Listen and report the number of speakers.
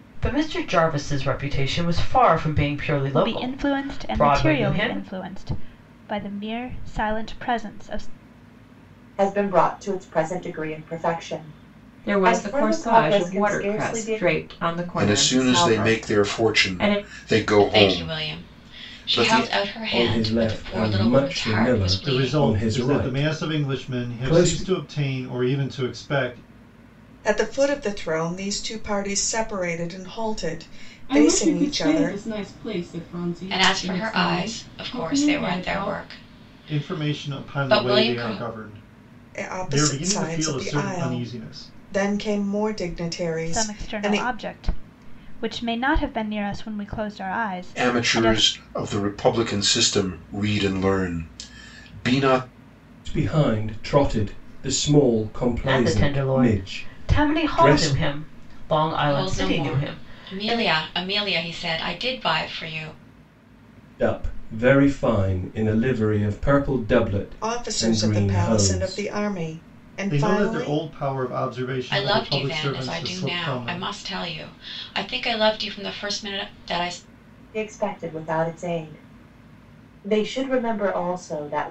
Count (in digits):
10